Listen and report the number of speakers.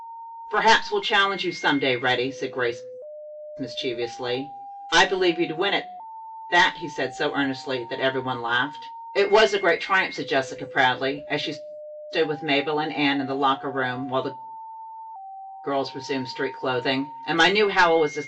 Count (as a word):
one